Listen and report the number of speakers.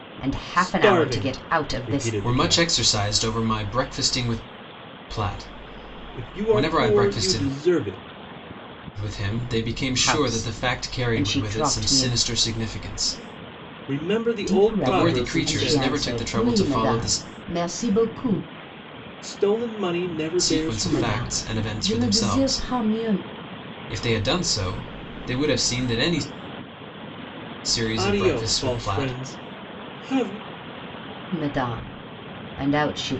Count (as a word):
three